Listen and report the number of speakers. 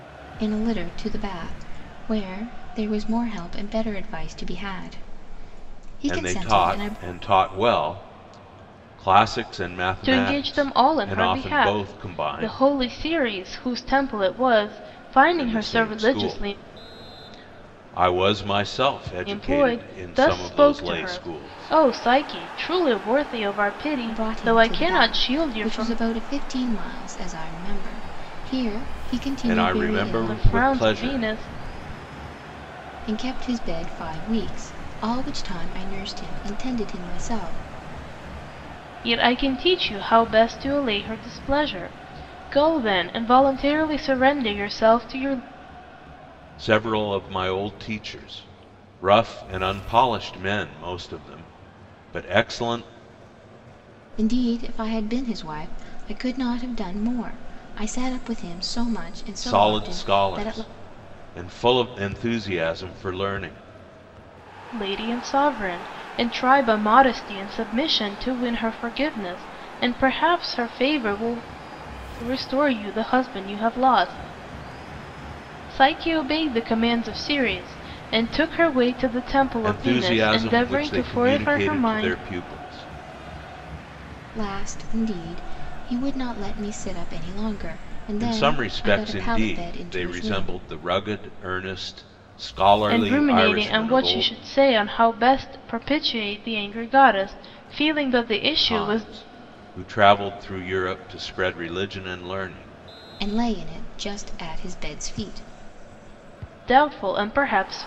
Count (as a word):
three